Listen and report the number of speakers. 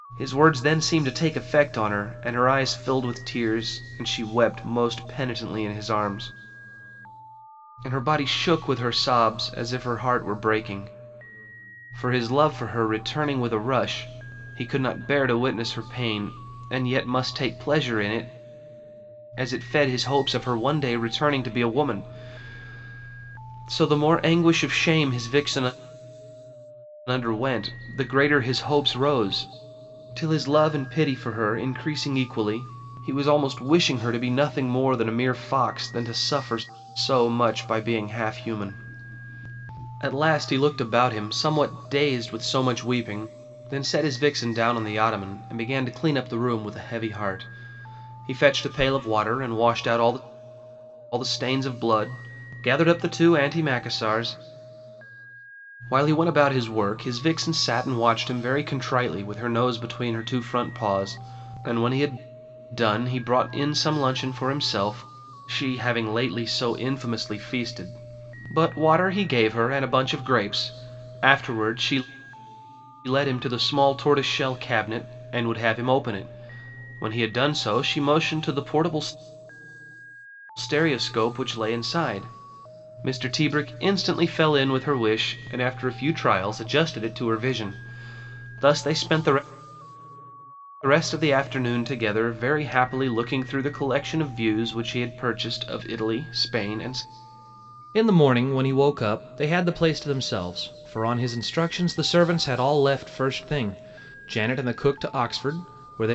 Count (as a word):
one